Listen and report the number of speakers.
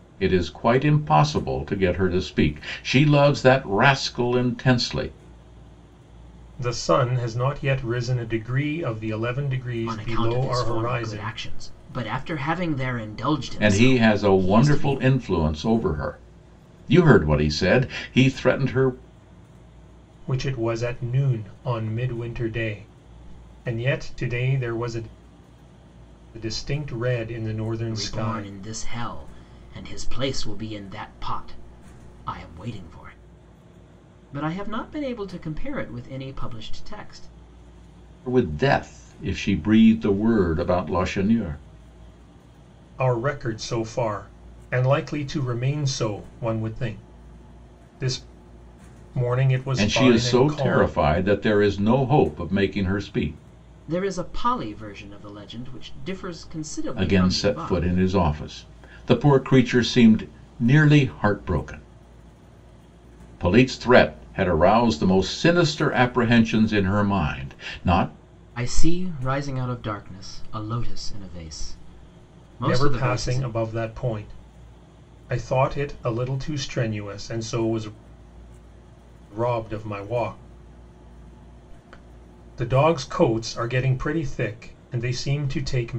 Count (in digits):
3